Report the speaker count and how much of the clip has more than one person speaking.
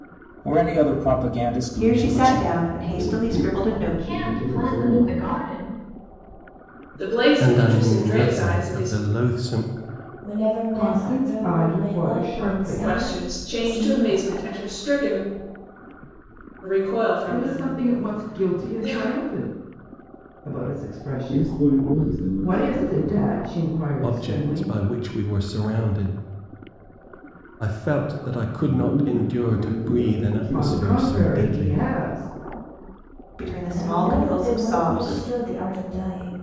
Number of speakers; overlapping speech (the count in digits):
8, about 49%